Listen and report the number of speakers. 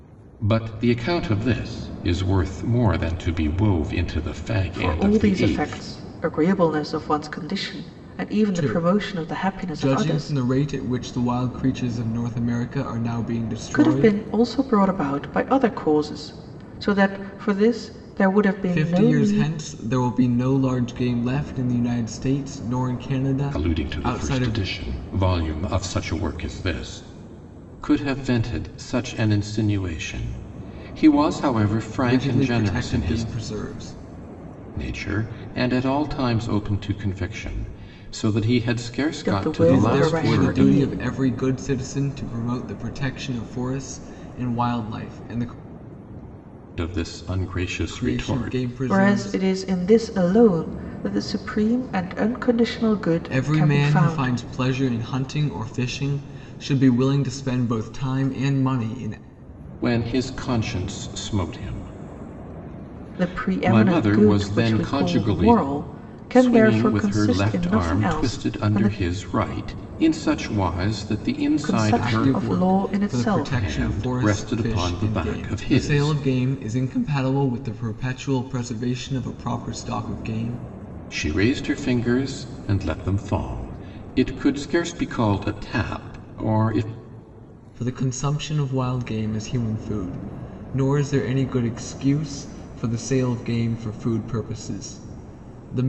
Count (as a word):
three